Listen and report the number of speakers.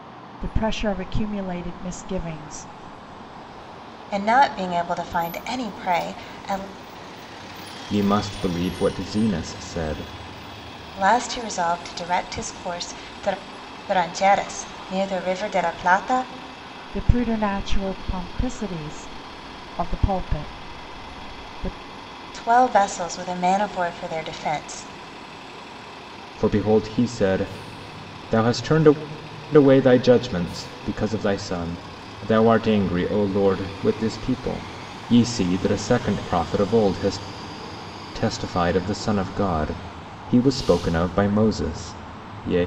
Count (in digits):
3